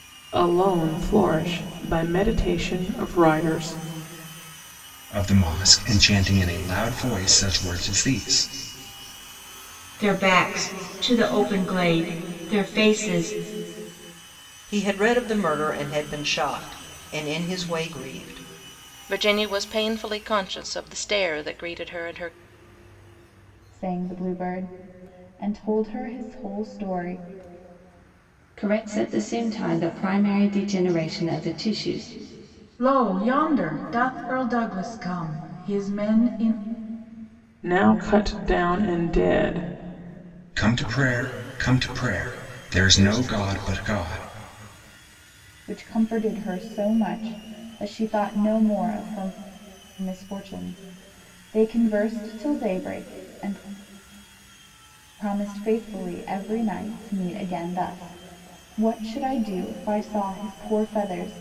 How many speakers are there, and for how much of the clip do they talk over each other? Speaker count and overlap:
8, no overlap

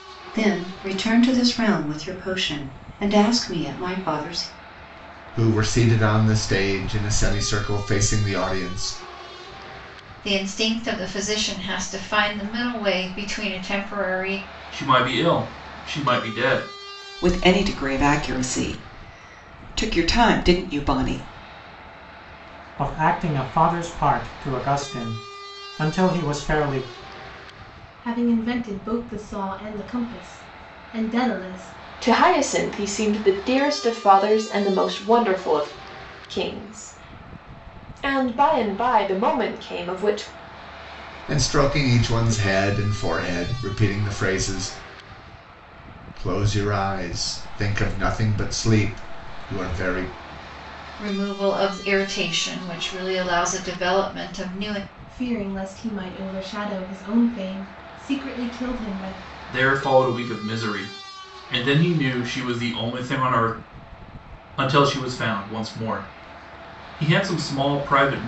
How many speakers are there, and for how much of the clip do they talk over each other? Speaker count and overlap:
8, no overlap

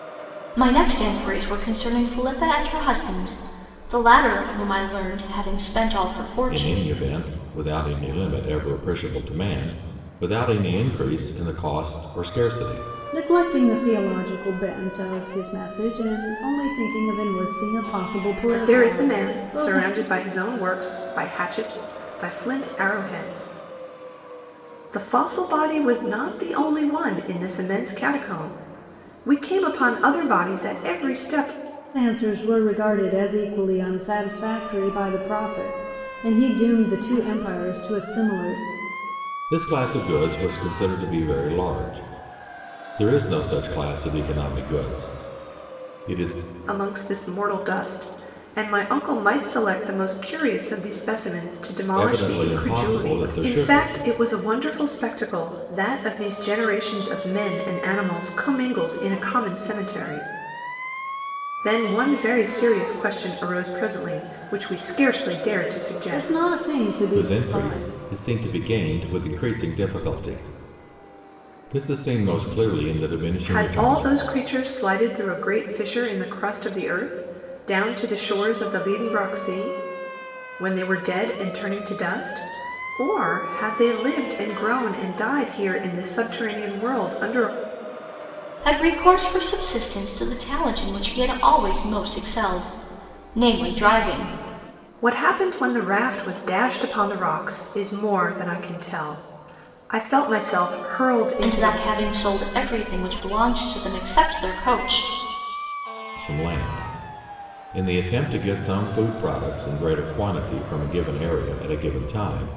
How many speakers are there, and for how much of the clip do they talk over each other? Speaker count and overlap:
4, about 6%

